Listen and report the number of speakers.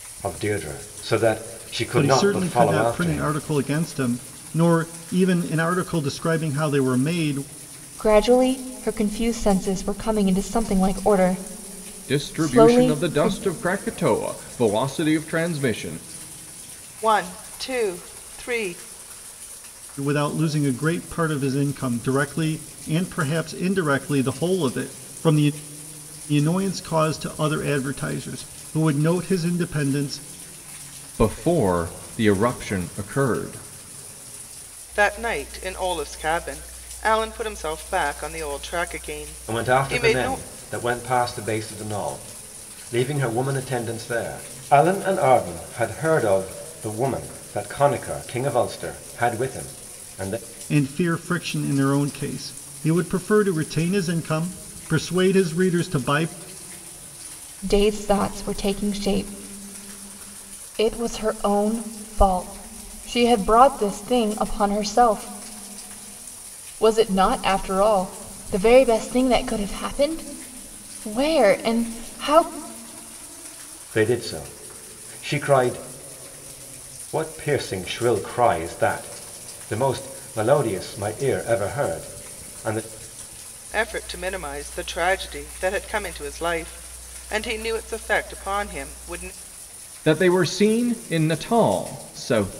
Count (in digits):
5